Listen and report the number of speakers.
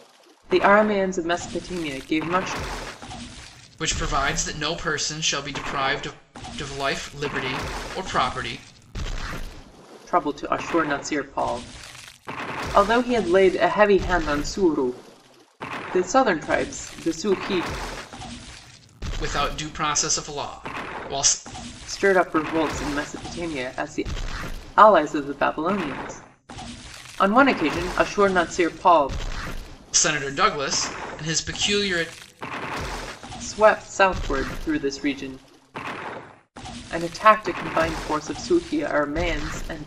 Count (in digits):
2